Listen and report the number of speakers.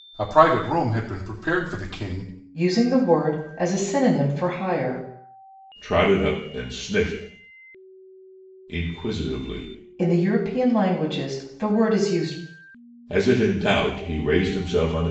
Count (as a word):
three